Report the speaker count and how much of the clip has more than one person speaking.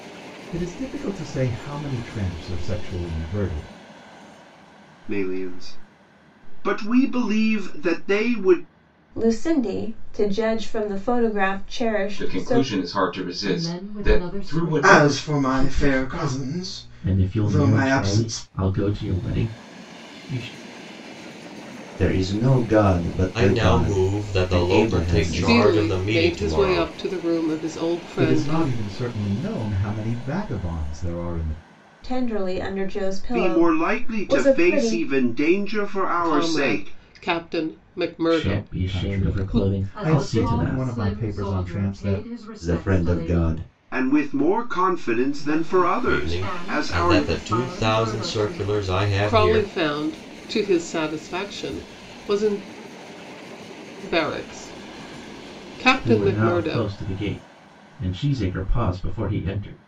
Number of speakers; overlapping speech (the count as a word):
ten, about 36%